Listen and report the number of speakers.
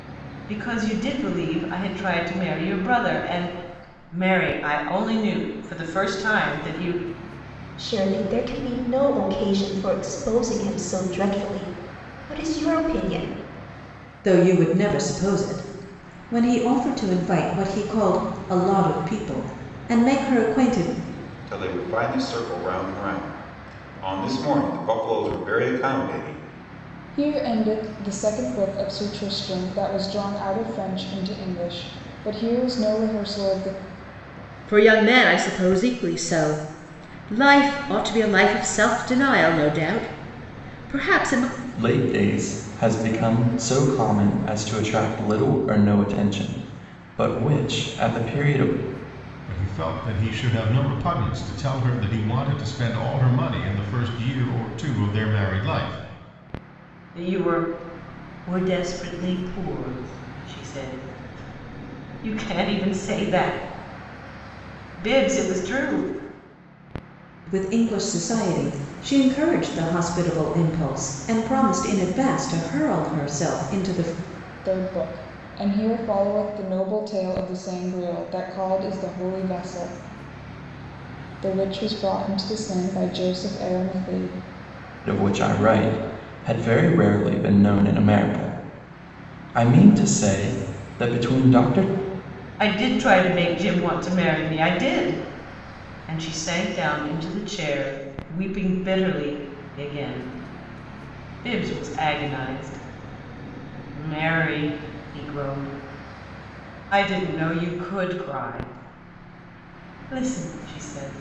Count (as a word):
eight